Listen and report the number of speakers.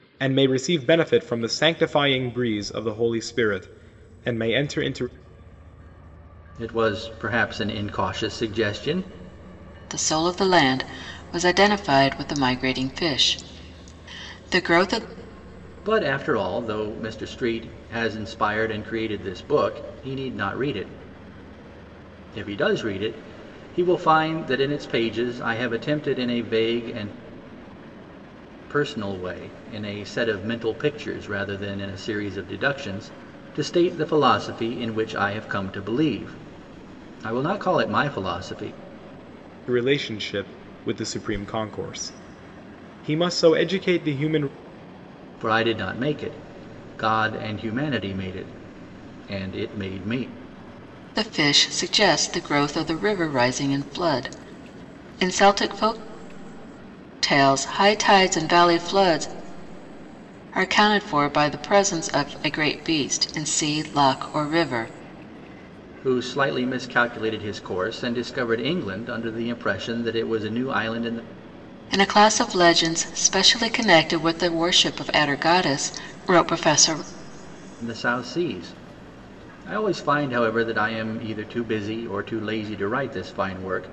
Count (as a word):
three